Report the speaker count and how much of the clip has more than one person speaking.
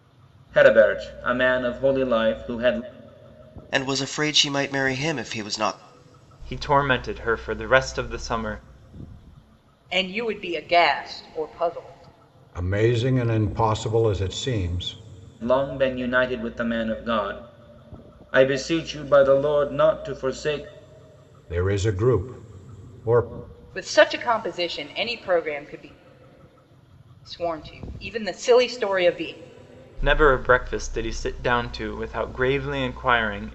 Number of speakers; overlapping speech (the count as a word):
five, no overlap